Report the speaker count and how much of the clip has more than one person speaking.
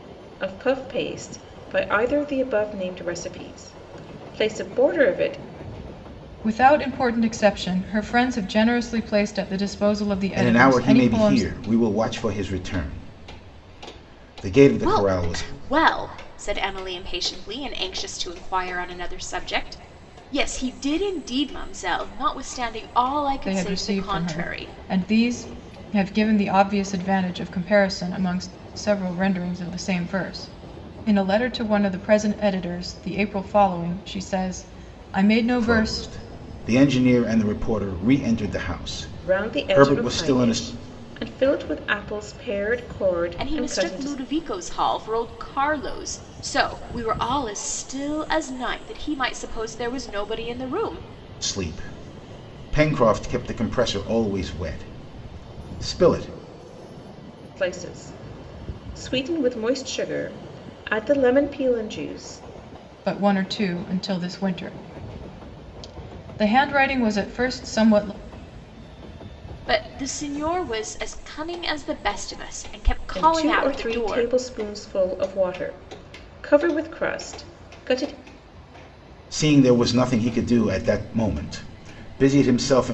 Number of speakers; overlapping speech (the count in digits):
4, about 9%